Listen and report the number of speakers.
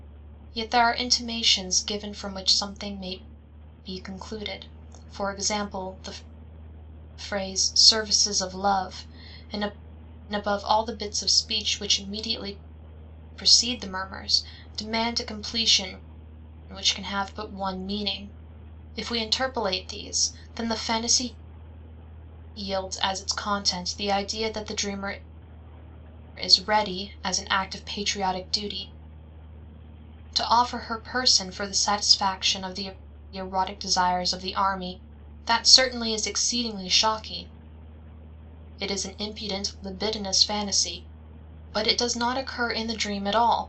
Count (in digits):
1